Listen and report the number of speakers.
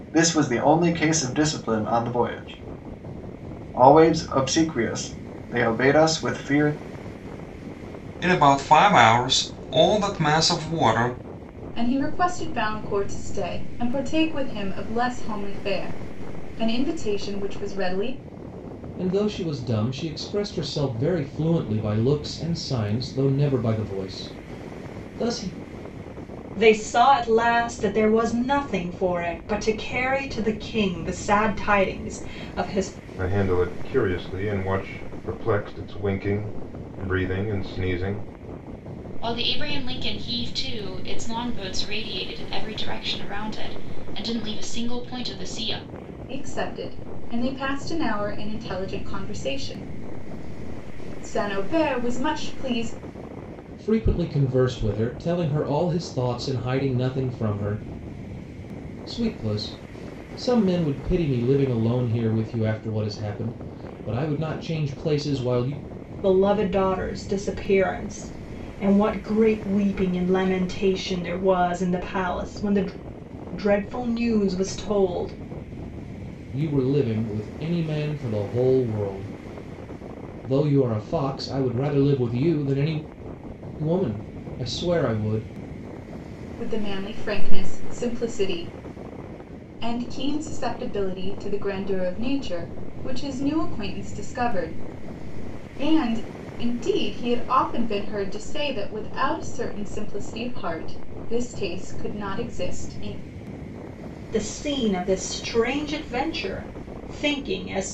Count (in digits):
7